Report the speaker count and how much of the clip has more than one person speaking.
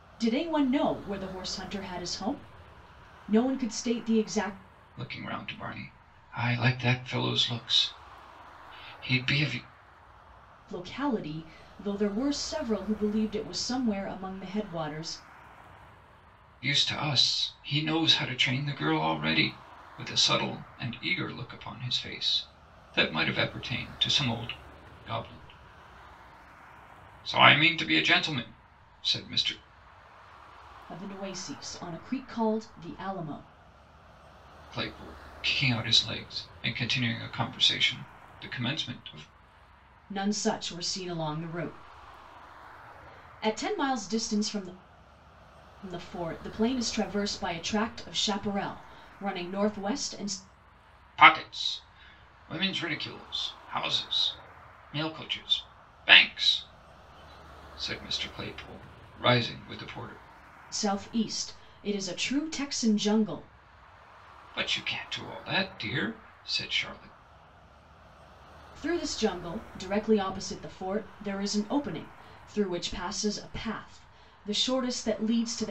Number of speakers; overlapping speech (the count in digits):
2, no overlap